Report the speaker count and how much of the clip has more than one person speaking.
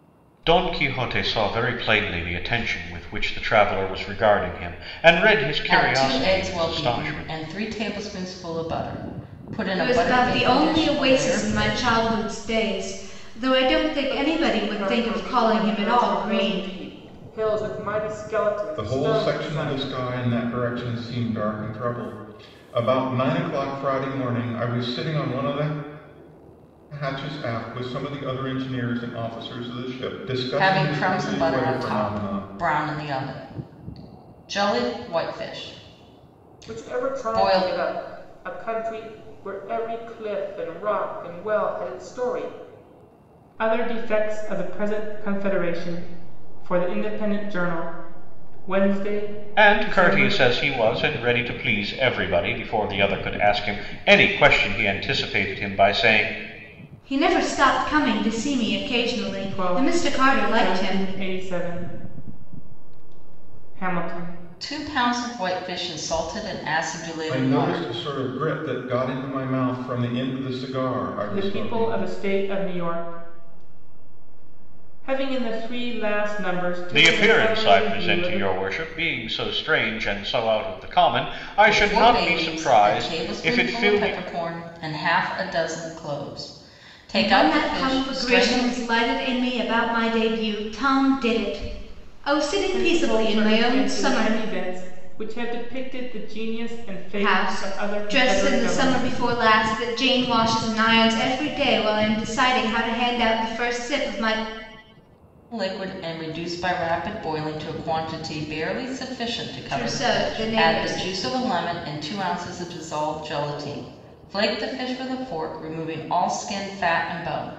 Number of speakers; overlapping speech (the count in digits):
5, about 22%